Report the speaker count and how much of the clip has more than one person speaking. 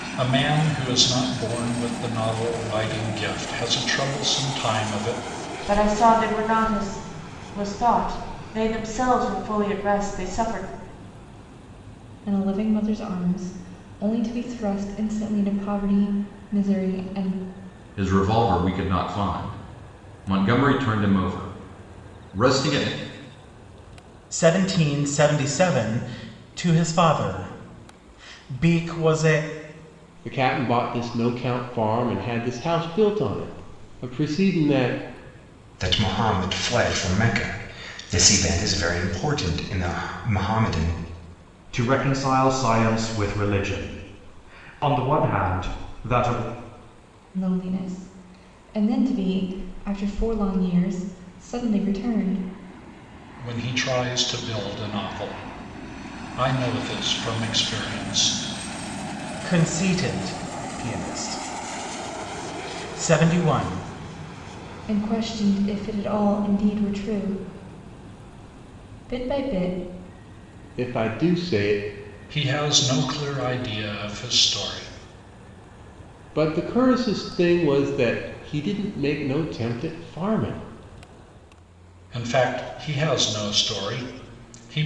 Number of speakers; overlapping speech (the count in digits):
8, no overlap